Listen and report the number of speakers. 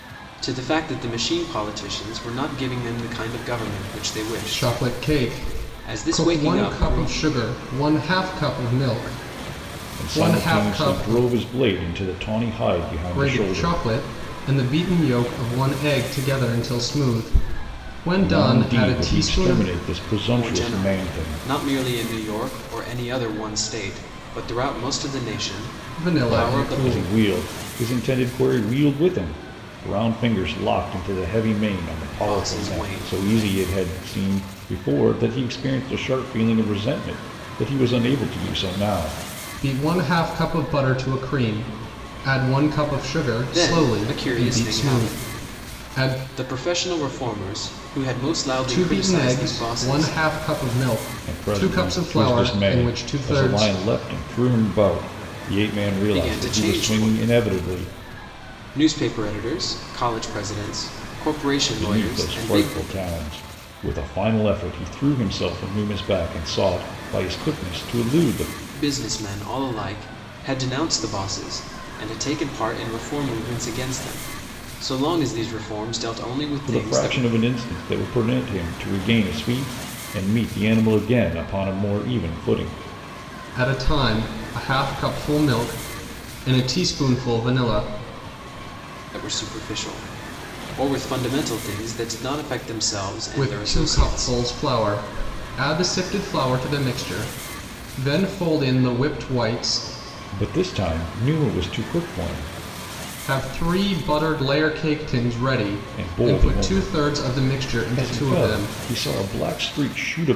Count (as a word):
three